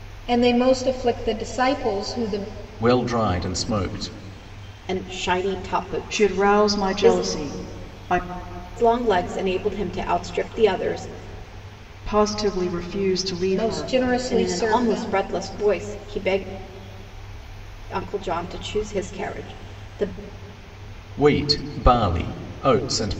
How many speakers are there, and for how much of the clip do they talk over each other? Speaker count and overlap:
4, about 11%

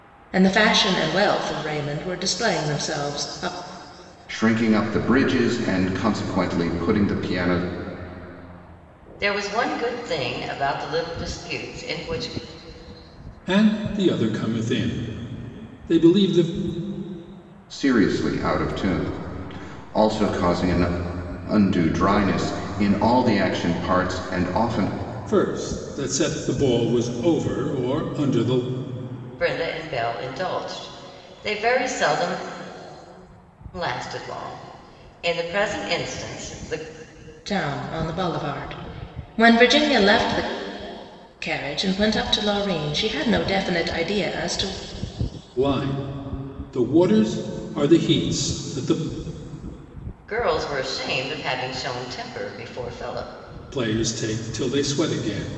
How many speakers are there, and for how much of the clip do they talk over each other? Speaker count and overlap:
4, no overlap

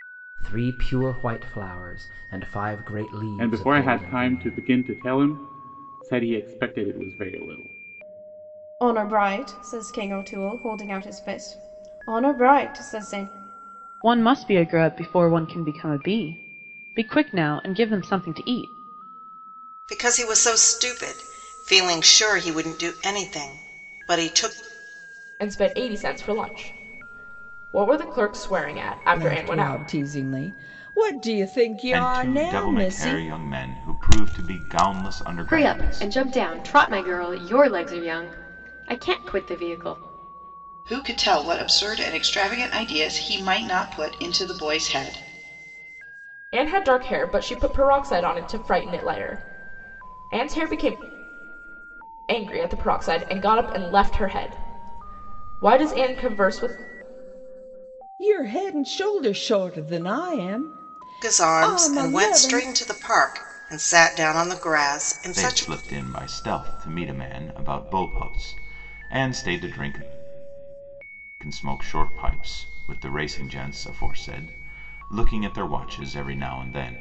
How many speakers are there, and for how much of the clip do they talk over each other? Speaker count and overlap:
10, about 8%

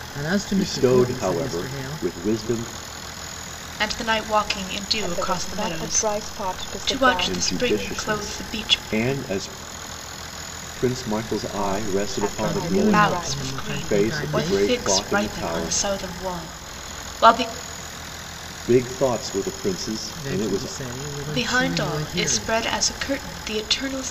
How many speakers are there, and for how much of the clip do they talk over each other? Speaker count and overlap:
4, about 45%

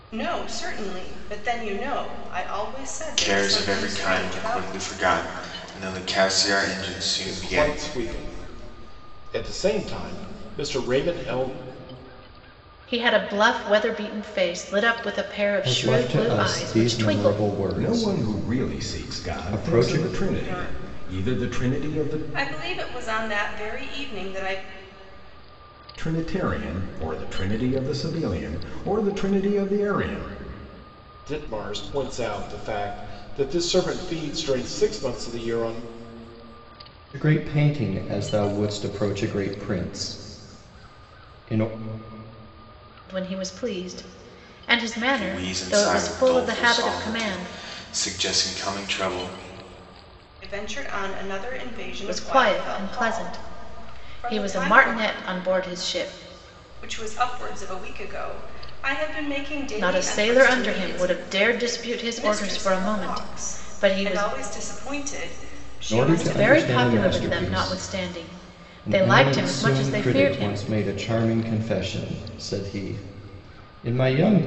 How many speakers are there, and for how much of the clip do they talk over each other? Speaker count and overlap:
6, about 28%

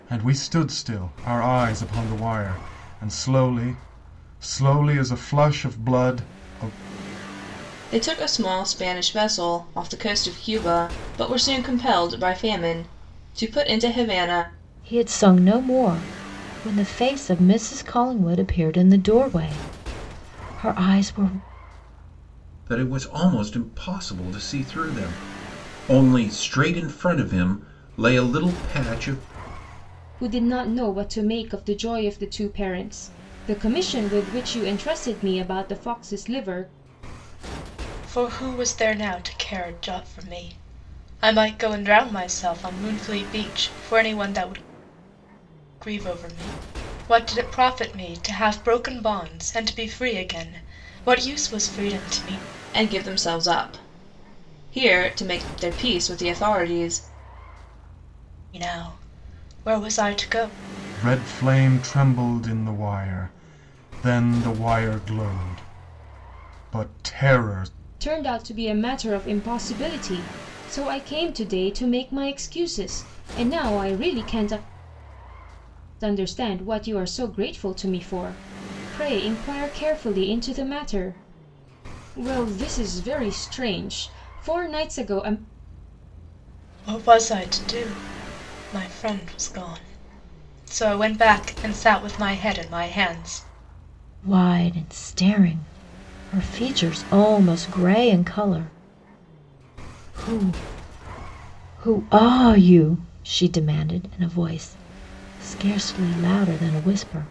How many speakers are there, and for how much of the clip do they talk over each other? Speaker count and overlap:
6, no overlap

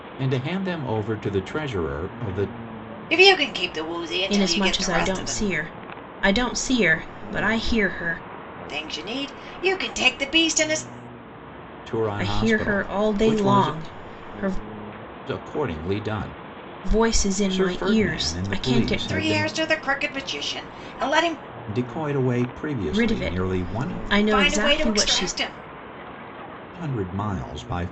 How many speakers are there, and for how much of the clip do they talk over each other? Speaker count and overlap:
3, about 25%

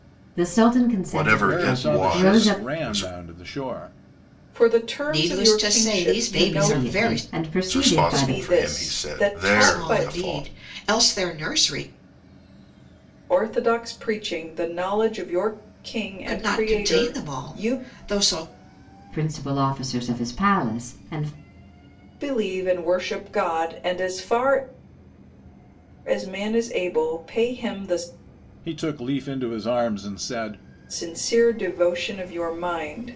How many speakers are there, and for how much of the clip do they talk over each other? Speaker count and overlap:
5, about 26%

